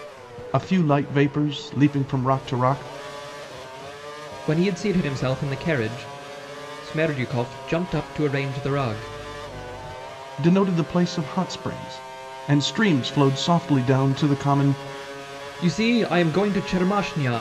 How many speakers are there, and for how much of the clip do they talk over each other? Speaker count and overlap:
2, no overlap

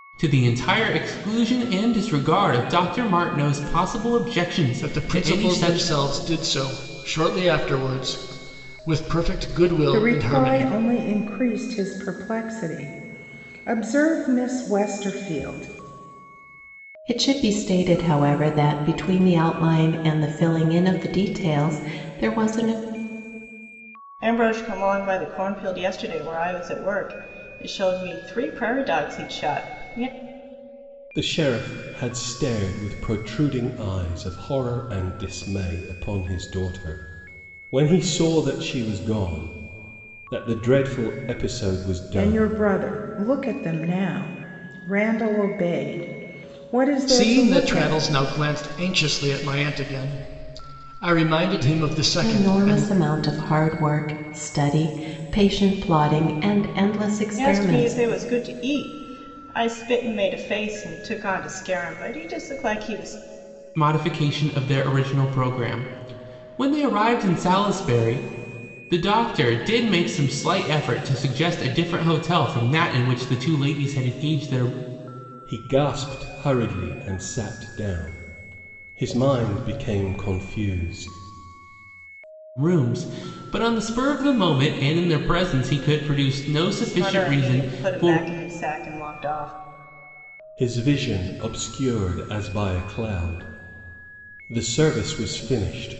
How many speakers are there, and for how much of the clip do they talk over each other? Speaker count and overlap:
6, about 6%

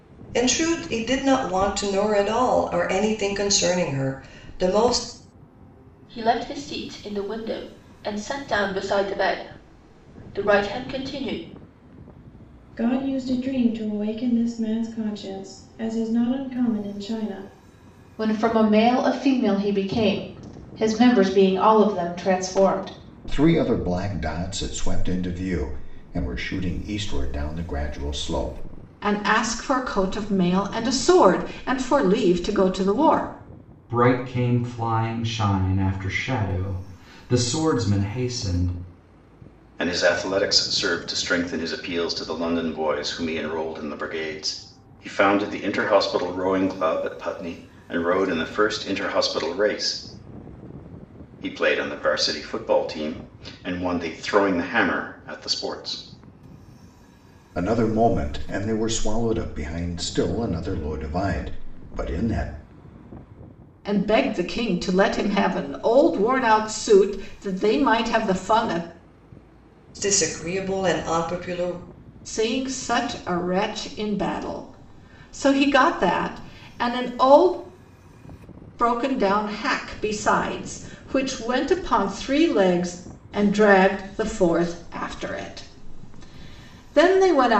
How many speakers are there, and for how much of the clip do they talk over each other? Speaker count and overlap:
8, no overlap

